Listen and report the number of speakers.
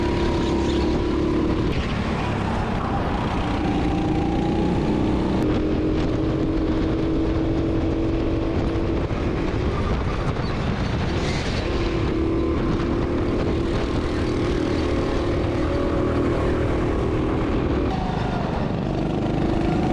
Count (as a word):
zero